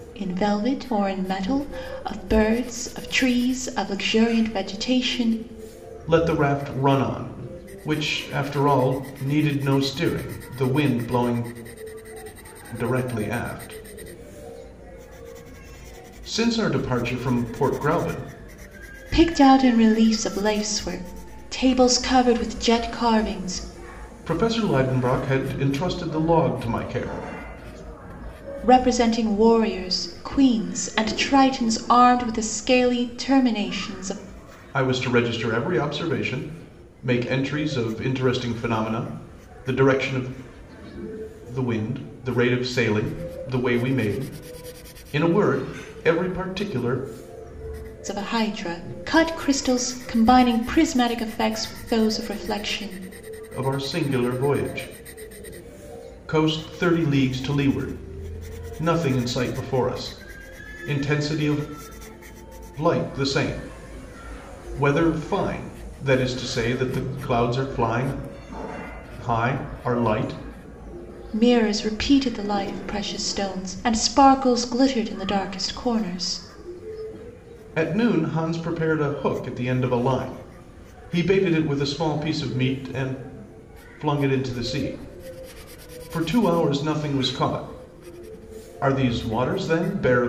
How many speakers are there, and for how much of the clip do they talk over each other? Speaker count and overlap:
2, no overlap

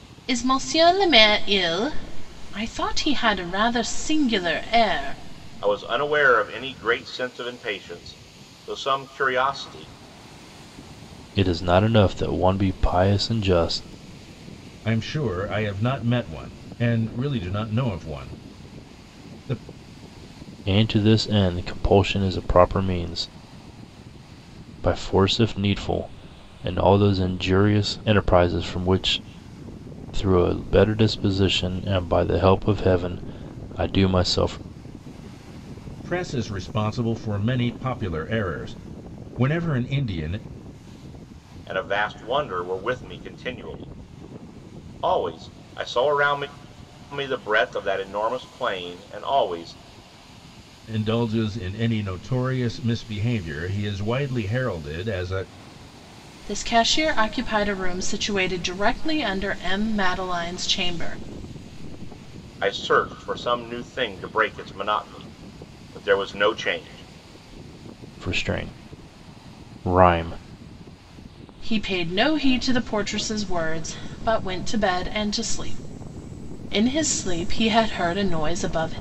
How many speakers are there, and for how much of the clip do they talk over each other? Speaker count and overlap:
4, no overlap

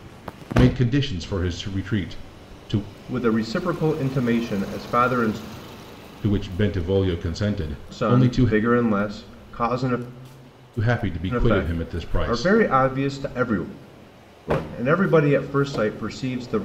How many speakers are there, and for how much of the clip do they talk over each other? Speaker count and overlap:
2, about 11%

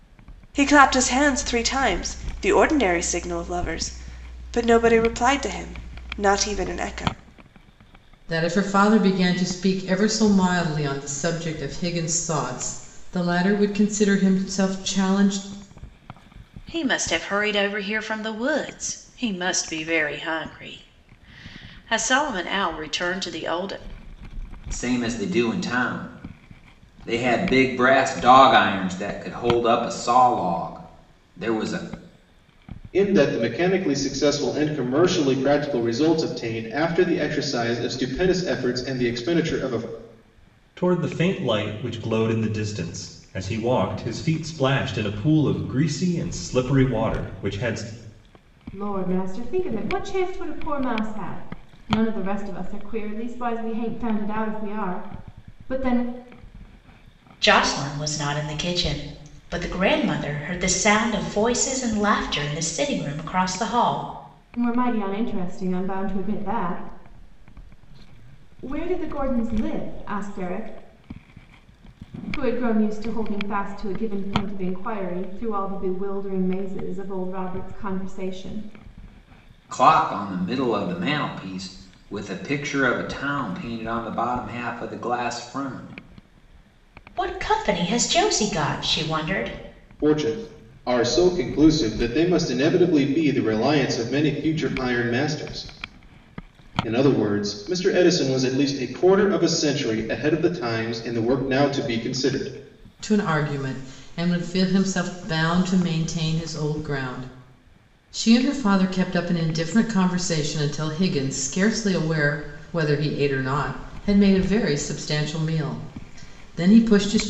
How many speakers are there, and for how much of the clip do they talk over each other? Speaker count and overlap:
8, no overlap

